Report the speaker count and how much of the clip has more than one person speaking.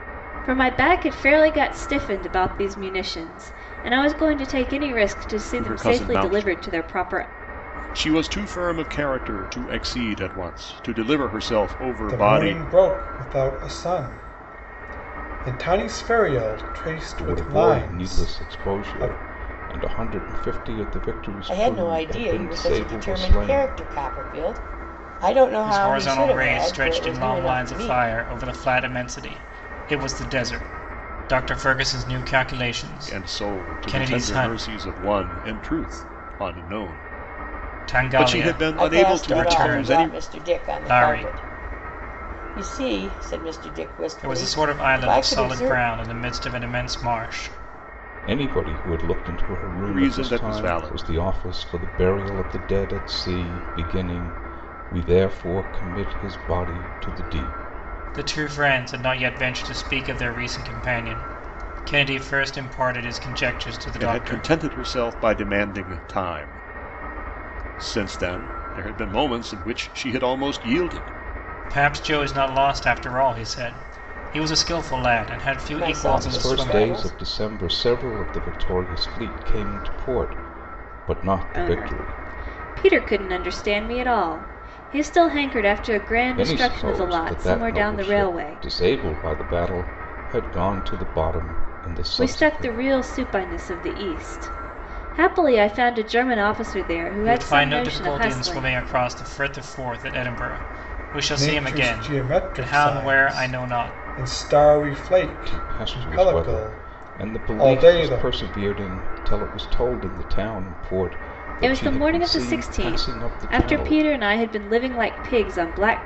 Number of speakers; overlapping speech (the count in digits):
6, about 28%